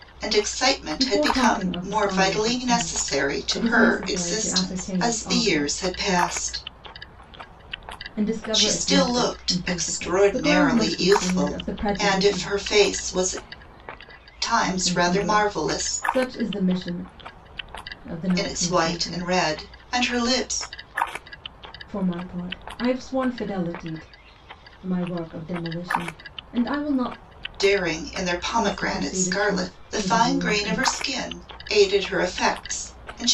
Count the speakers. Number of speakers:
2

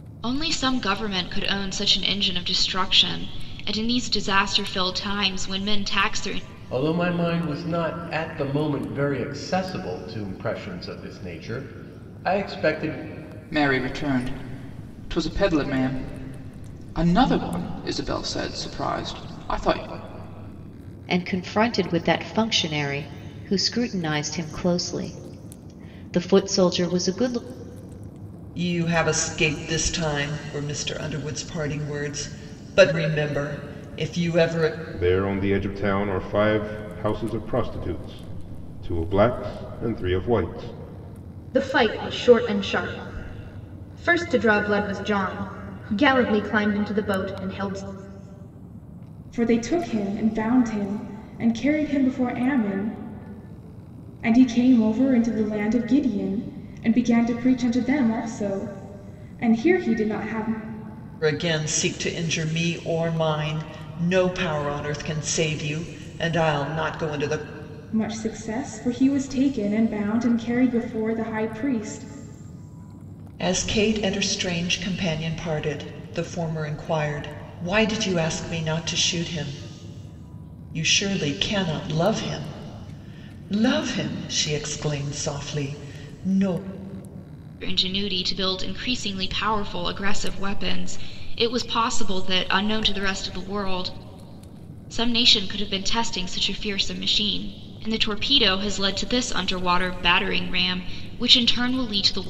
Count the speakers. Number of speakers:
8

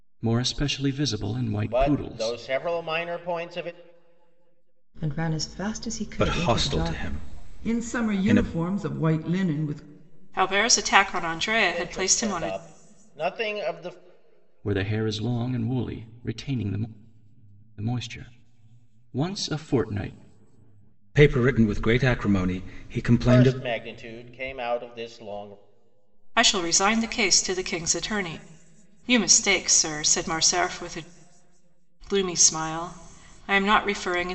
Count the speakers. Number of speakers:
6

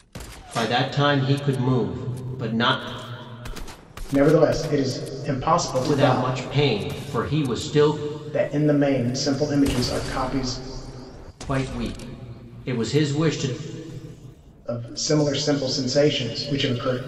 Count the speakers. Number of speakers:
2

